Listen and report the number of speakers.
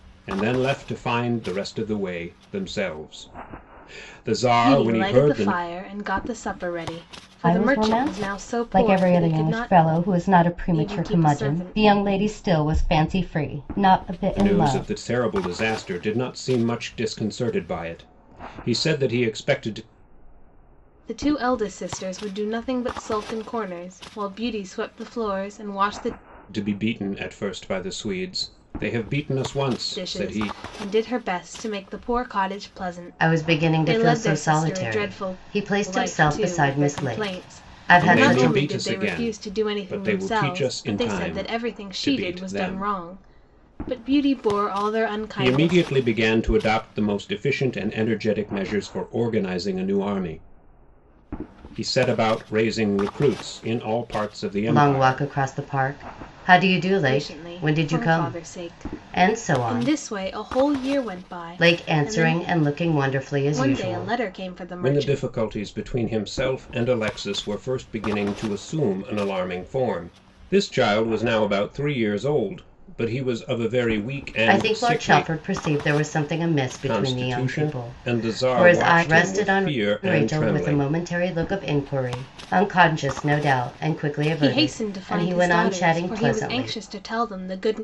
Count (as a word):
three